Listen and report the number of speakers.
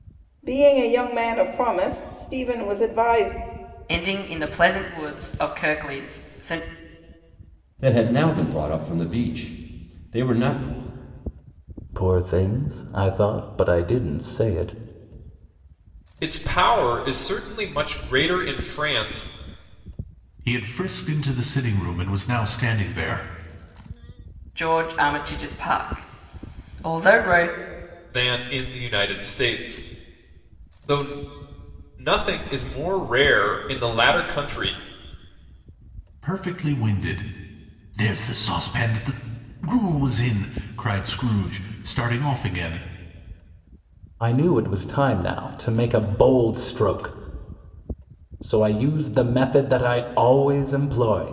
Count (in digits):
6